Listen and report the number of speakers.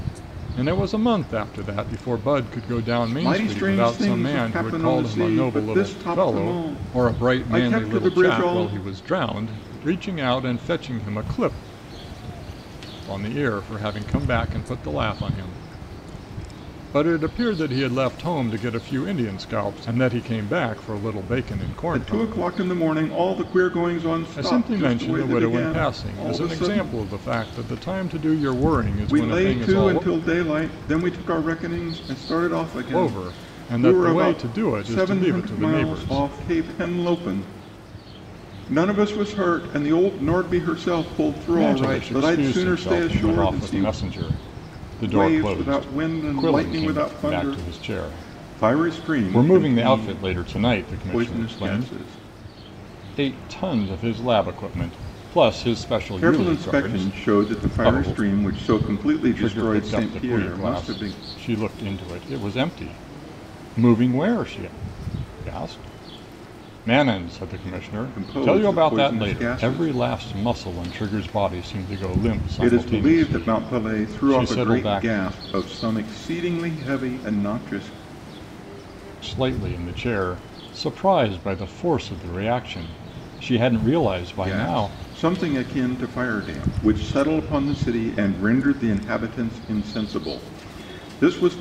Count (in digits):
2